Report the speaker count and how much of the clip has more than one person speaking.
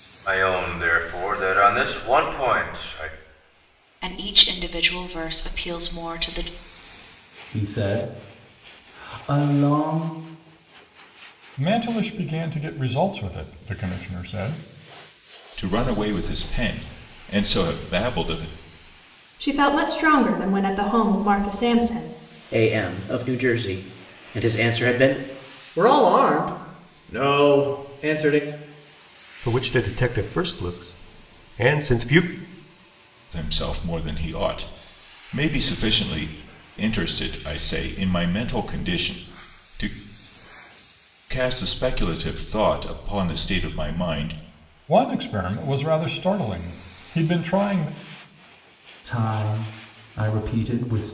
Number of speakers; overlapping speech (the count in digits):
9, no overlap